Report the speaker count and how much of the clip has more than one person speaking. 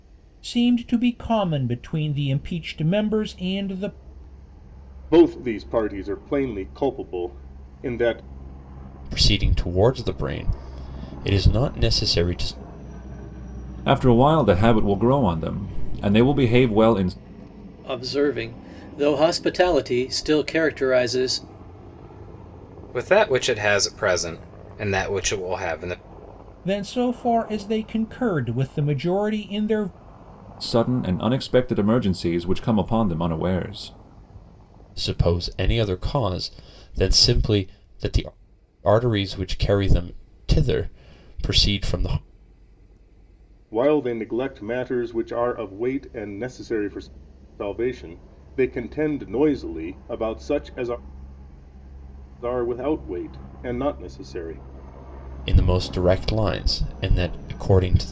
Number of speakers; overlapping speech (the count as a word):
six, no overlap